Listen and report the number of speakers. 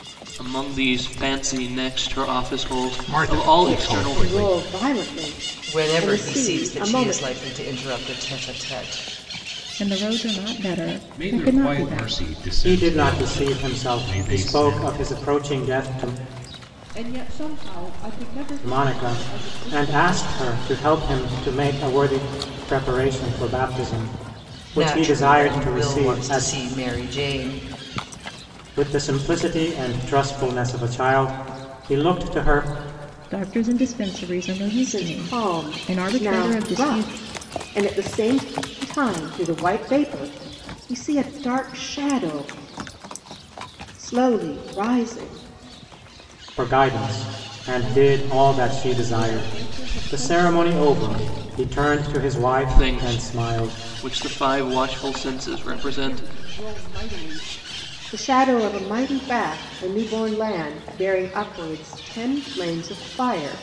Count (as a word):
eight